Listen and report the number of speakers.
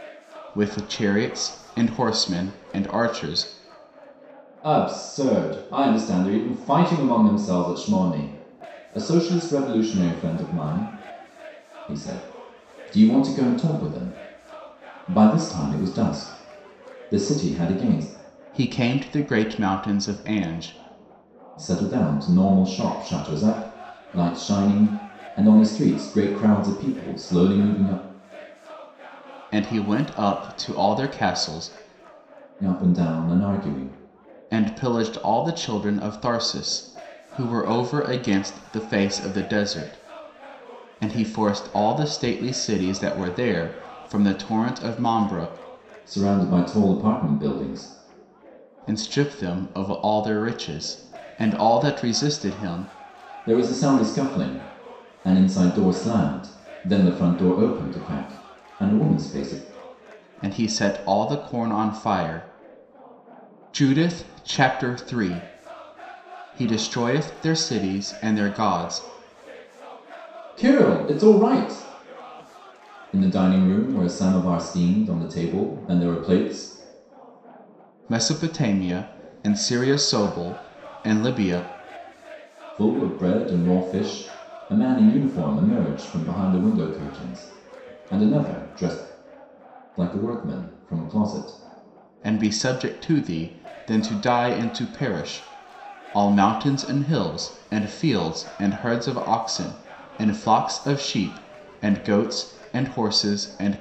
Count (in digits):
2